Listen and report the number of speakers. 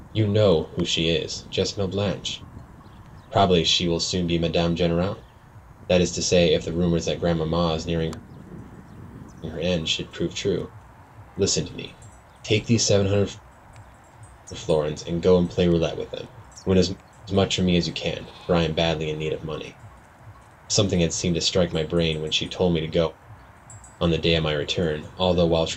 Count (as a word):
one